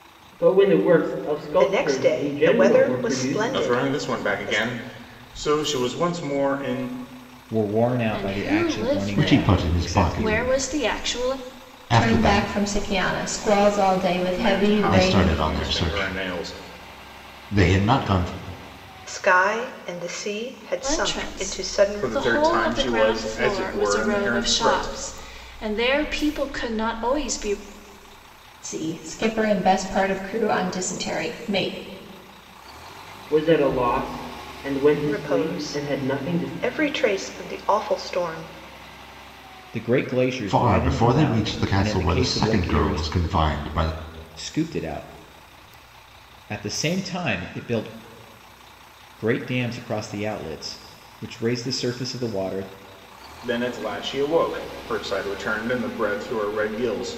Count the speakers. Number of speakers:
seven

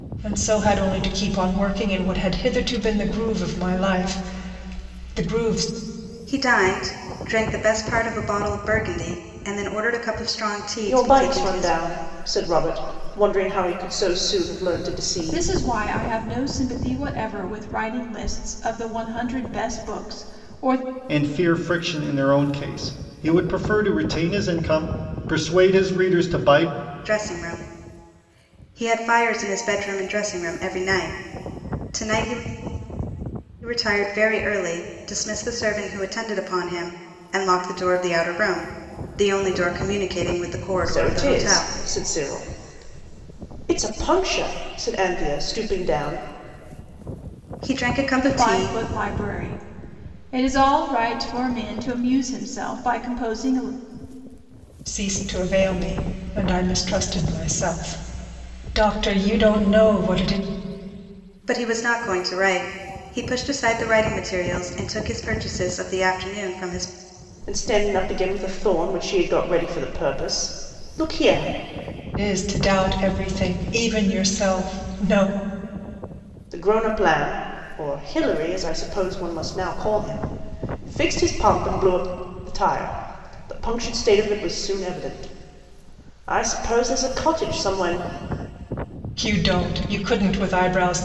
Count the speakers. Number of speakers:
five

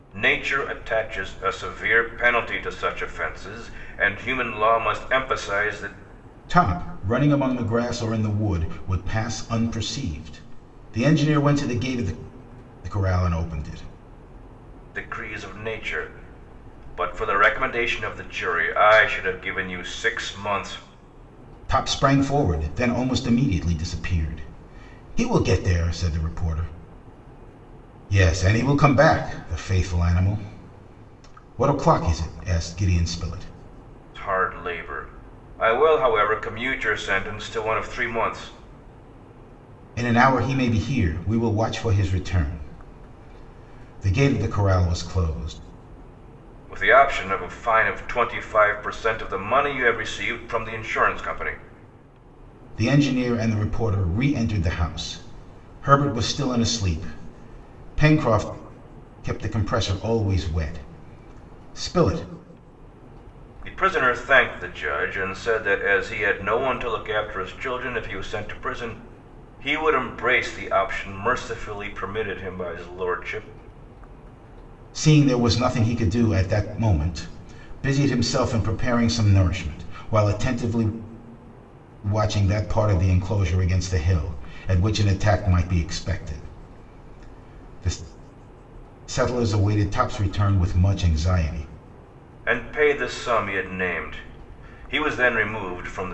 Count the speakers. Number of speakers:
two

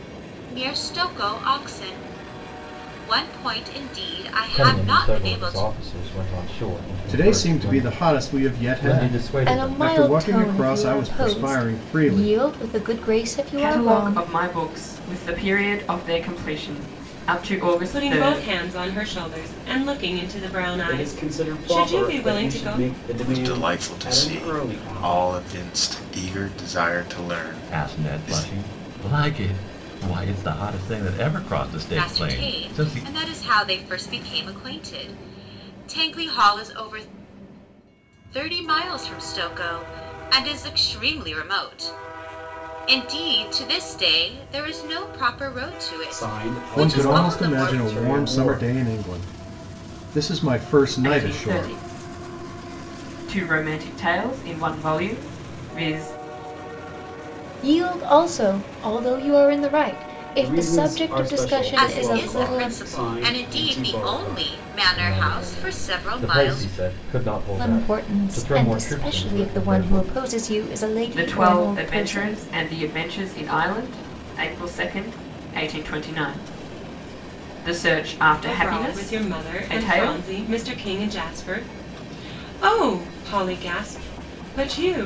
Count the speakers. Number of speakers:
nine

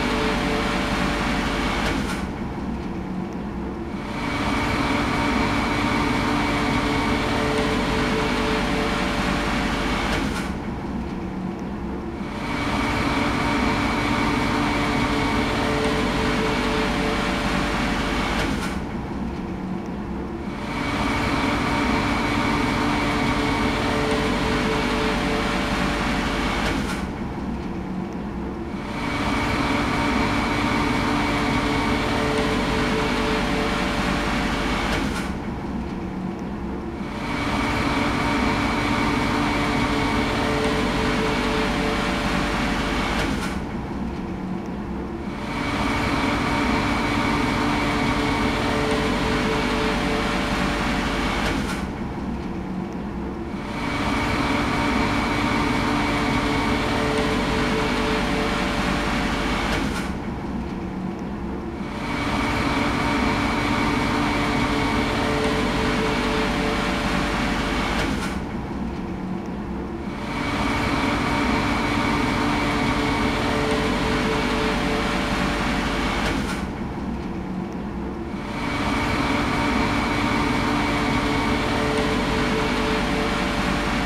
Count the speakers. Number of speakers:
zero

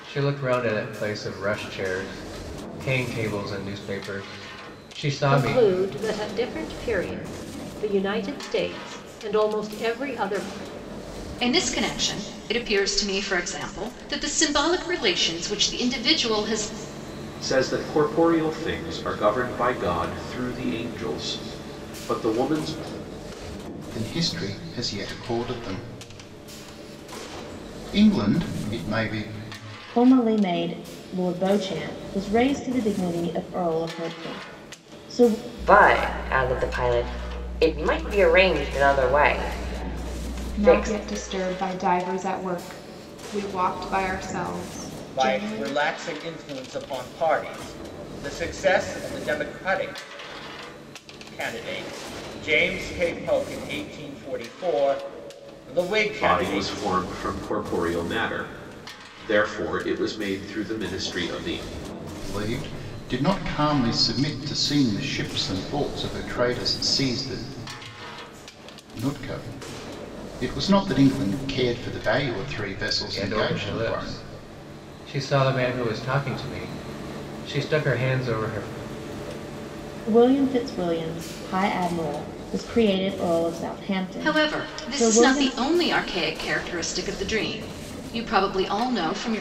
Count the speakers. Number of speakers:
nine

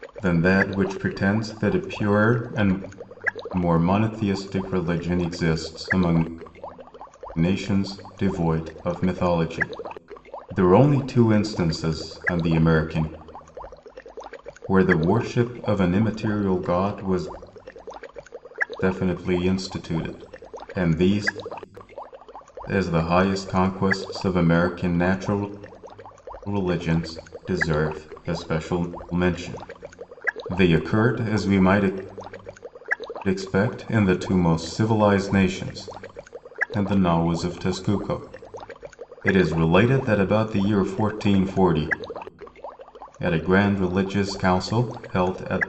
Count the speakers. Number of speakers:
one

